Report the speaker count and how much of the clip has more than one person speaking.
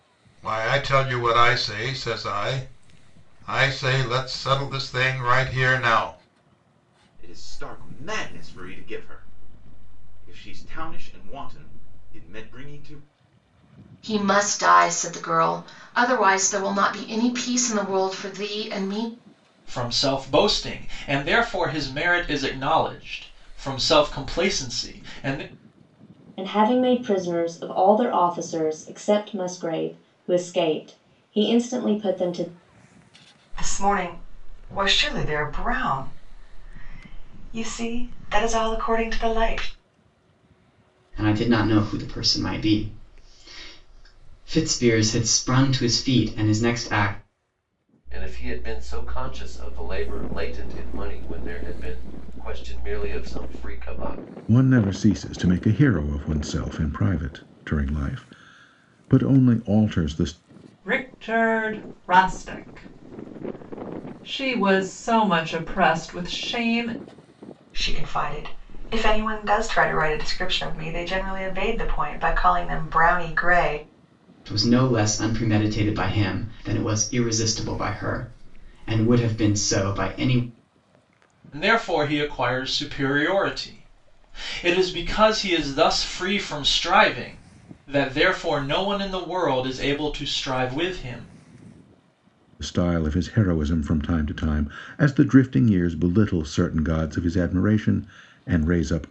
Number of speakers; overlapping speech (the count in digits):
10, no overlap